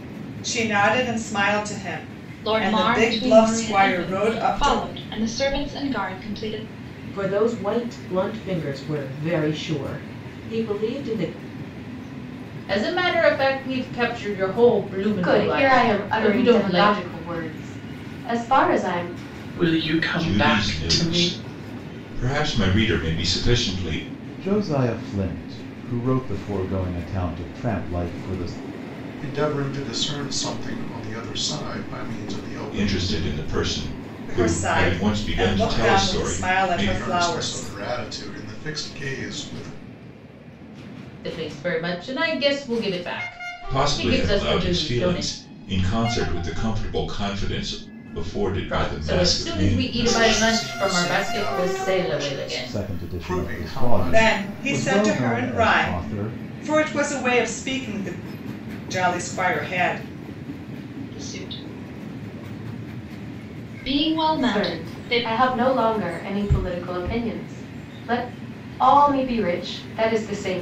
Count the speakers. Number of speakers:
9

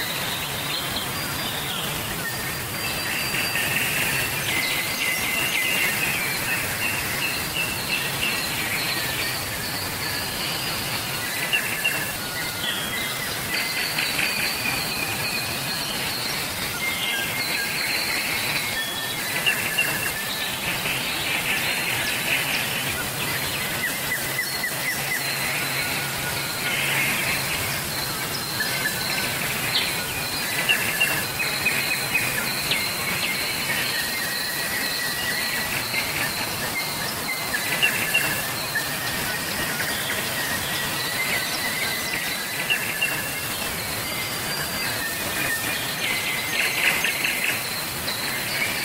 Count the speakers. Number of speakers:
0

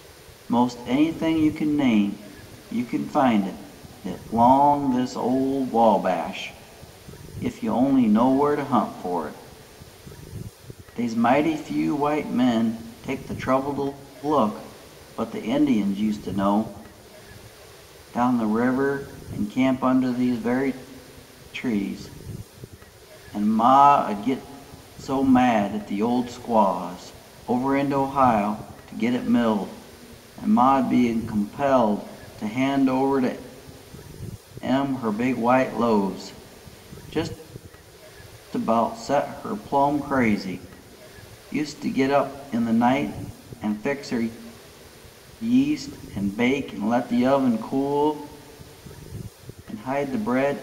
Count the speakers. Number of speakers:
1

